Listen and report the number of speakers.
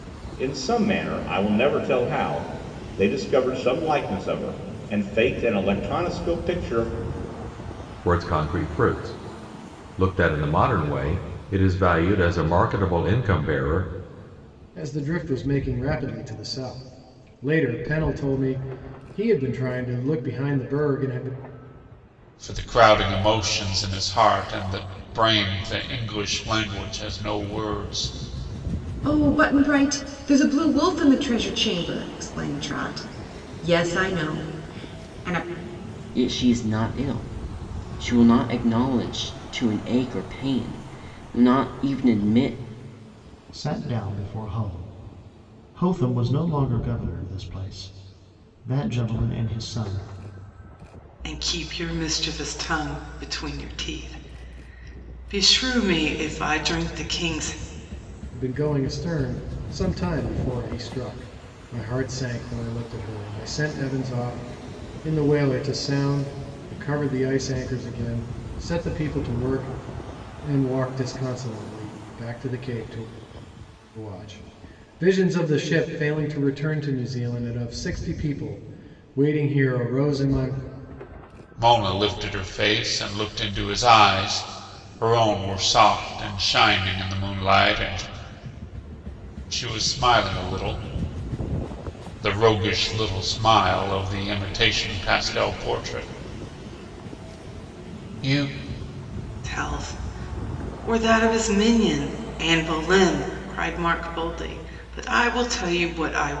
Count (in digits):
8